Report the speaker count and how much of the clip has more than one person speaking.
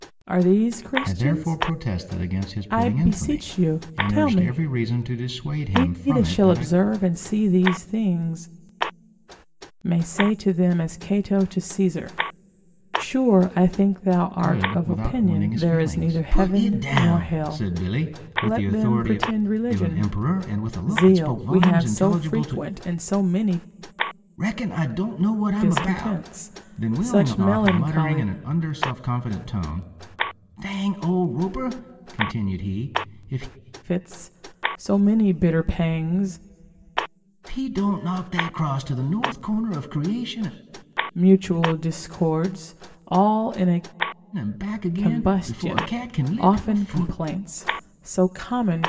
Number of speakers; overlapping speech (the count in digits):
2, about 35%